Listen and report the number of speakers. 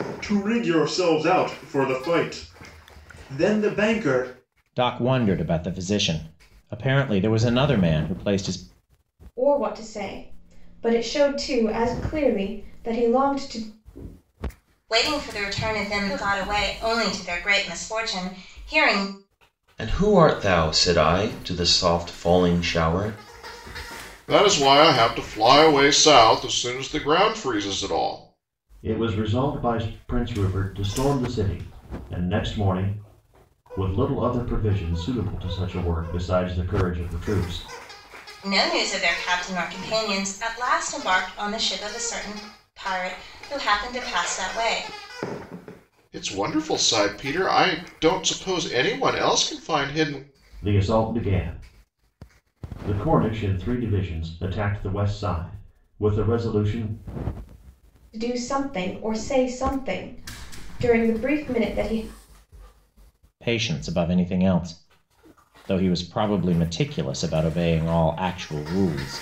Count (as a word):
seven